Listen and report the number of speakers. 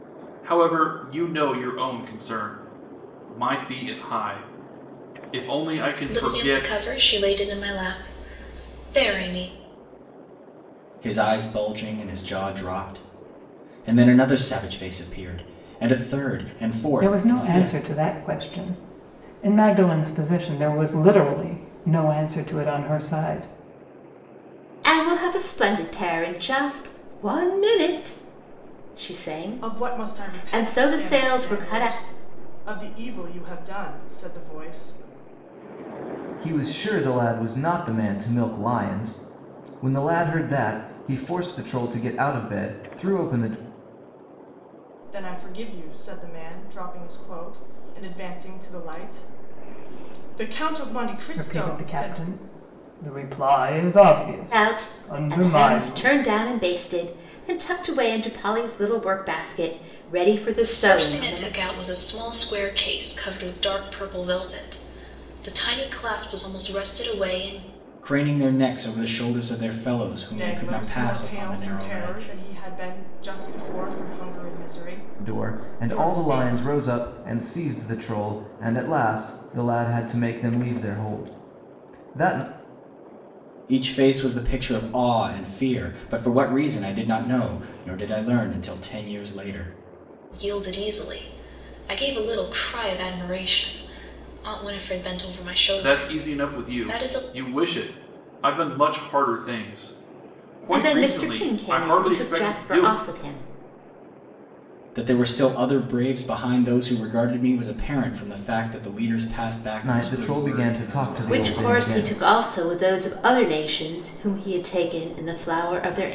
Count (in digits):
7